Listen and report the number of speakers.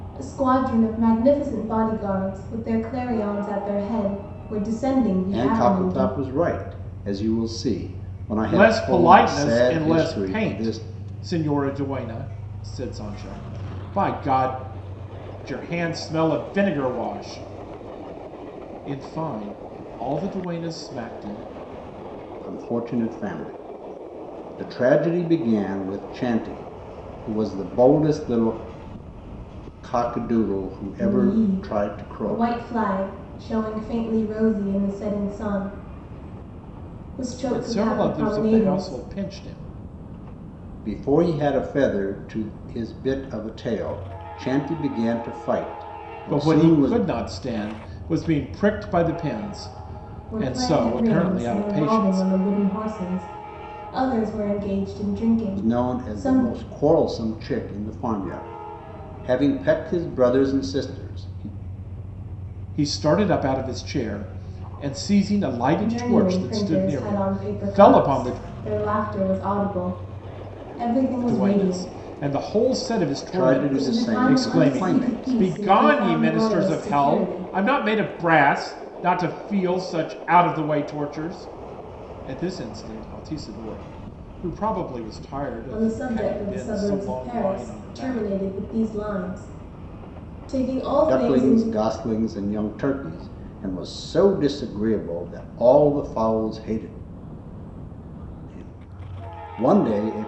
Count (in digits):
3